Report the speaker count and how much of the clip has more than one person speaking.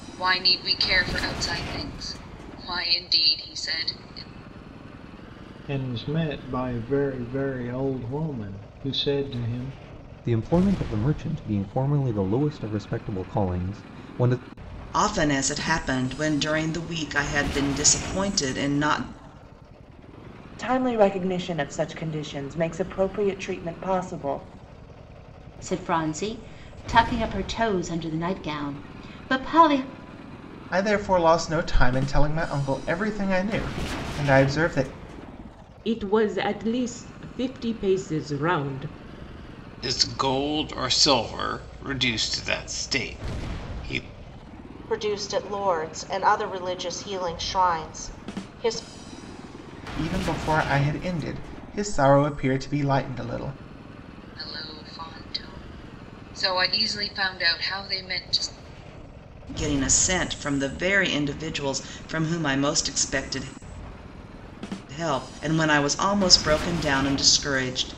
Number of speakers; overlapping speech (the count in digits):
10, no overlap